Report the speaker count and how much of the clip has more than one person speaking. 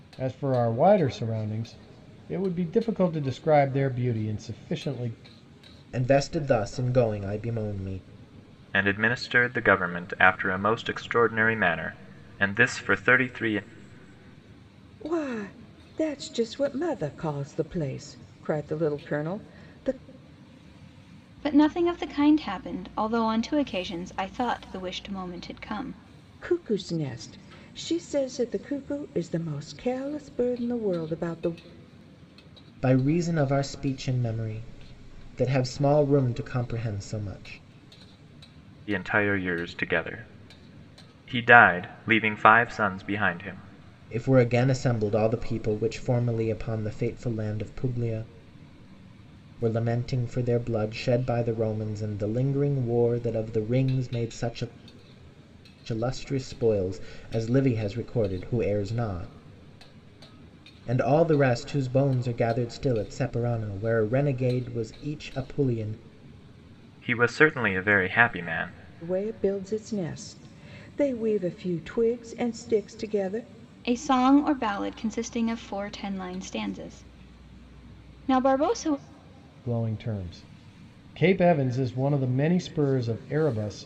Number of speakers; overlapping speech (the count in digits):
5, no overlap